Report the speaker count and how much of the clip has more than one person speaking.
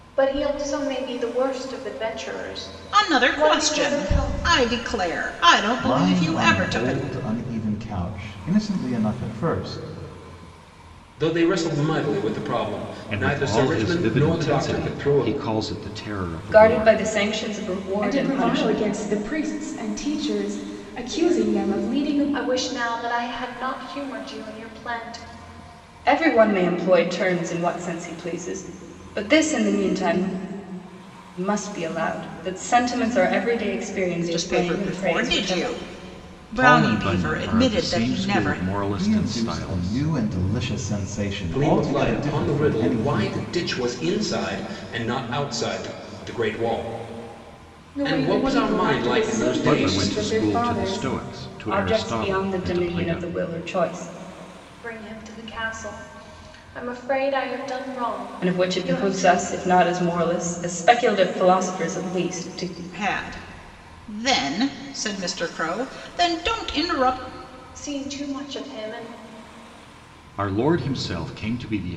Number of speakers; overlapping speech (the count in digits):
7, about 28%